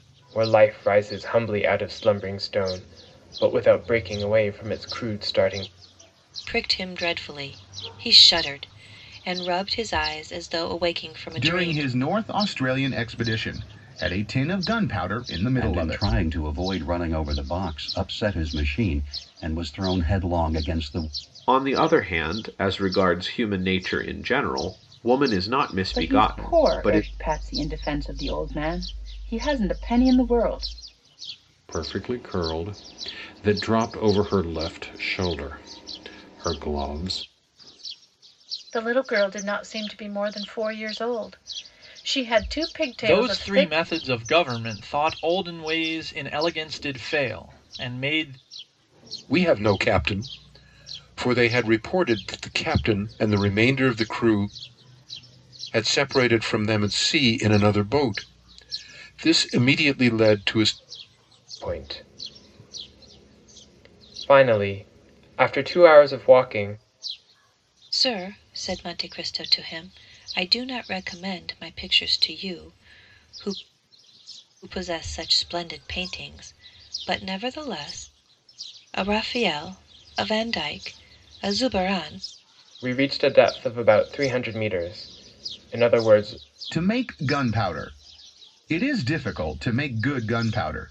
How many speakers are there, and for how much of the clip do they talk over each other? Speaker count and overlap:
ten, about 3%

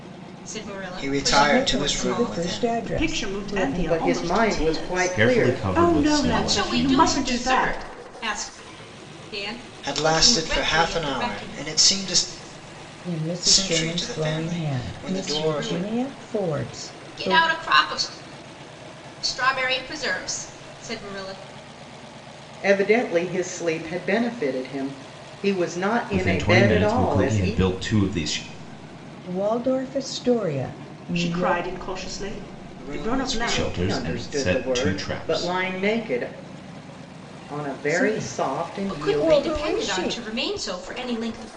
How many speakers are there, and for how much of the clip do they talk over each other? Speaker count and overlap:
six, about 47%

